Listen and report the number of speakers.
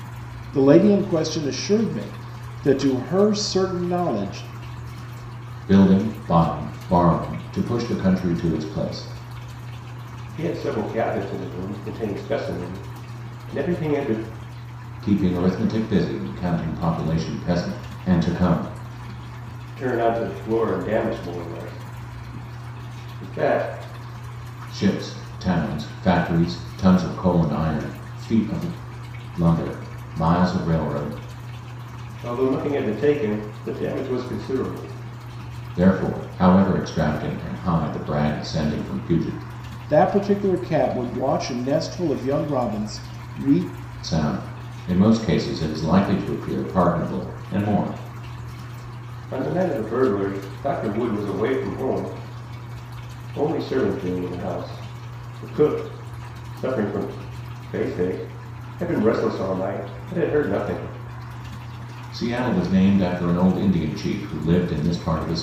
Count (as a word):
three